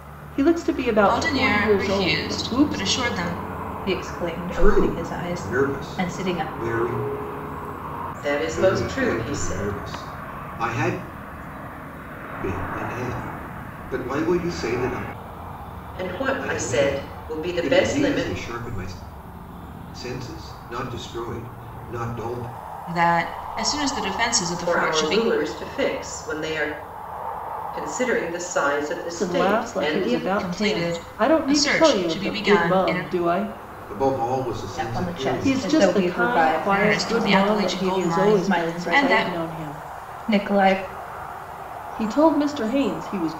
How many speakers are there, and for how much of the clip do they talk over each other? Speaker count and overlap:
5, about 38%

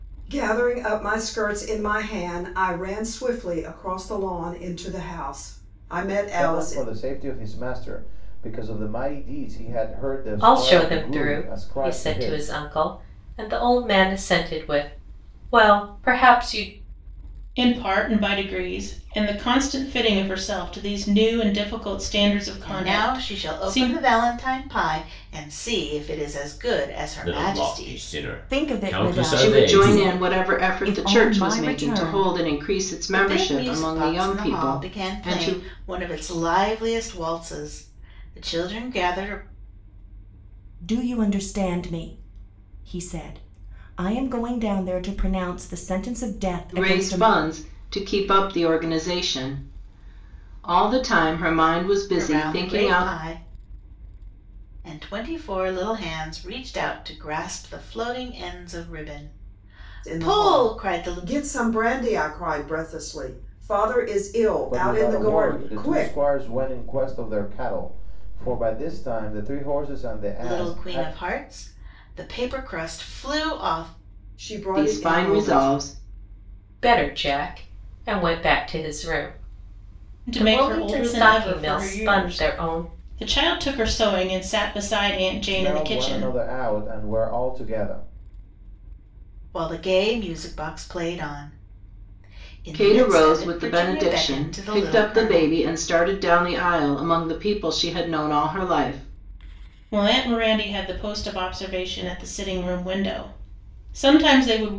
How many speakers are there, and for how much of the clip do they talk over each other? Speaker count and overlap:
8, about 23%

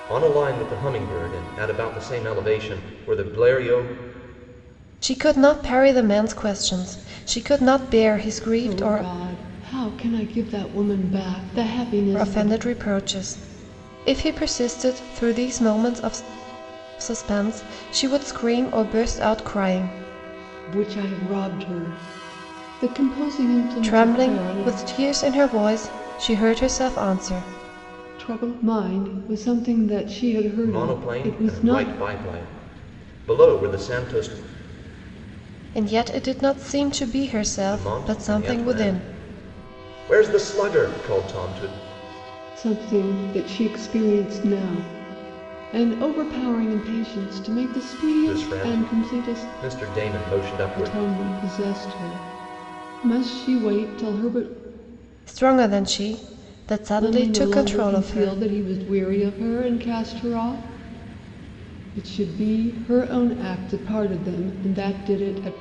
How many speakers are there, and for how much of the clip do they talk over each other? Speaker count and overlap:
3, about 12%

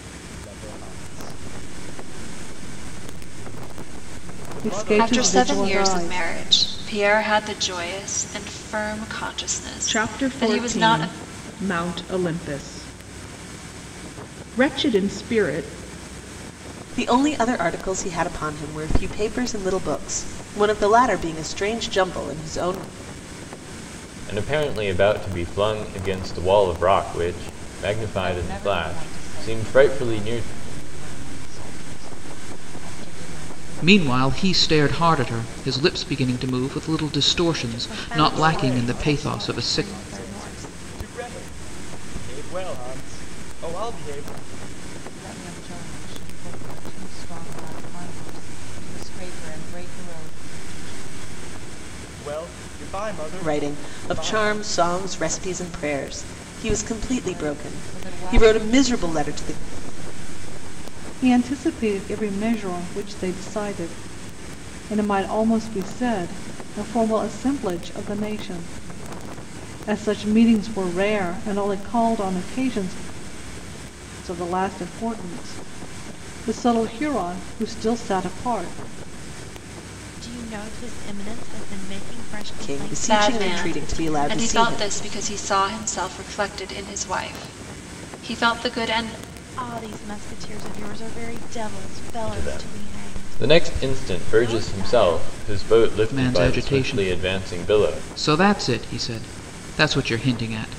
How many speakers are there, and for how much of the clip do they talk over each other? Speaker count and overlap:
9, about 21%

